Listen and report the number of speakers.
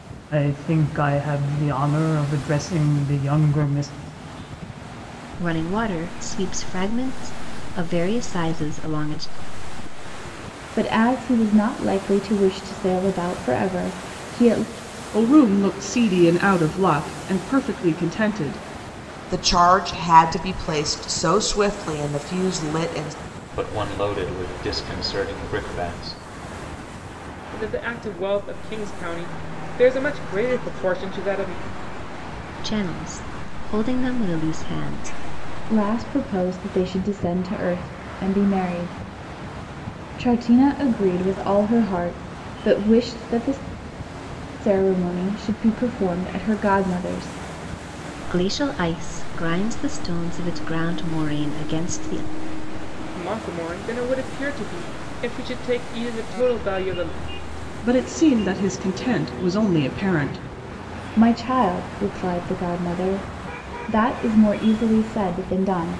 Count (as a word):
seven